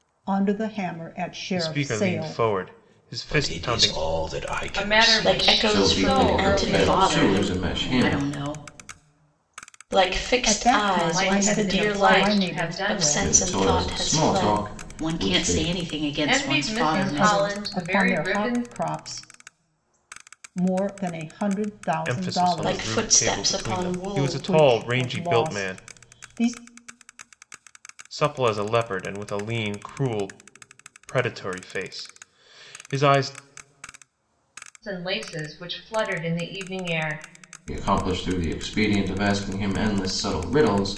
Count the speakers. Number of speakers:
7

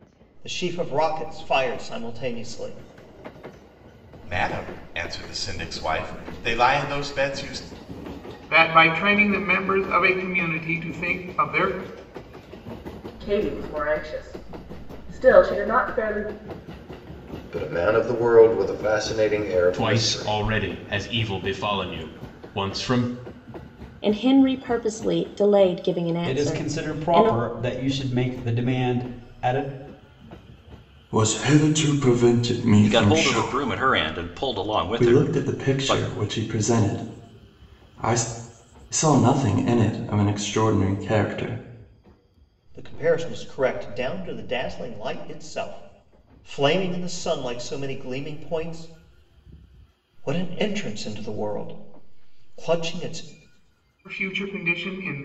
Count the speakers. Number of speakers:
10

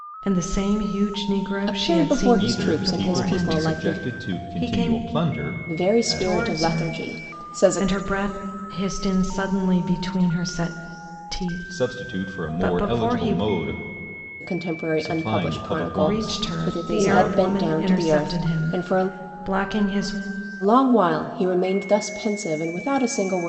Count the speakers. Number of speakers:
3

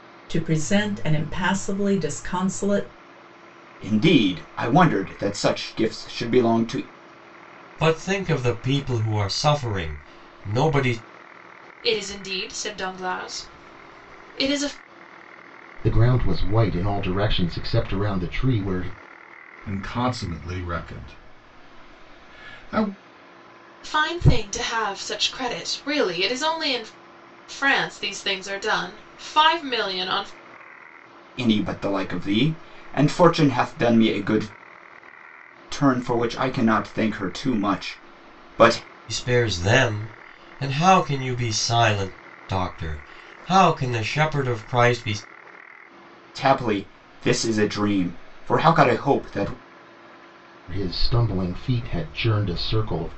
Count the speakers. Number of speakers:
6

